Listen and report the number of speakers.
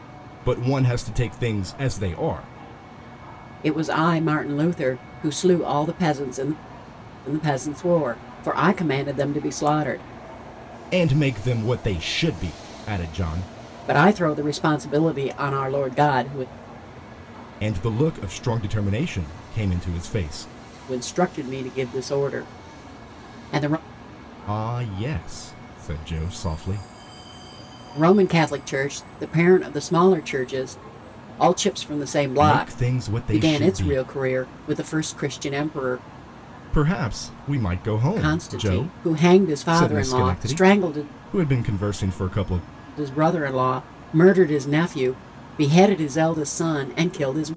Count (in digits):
2